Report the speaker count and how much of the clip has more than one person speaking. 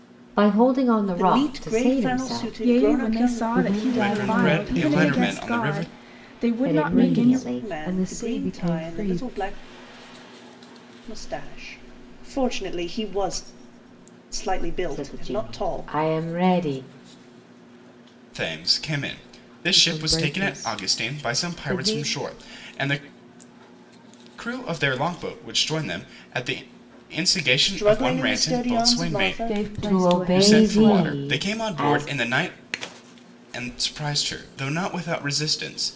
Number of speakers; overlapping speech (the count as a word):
five, about 43%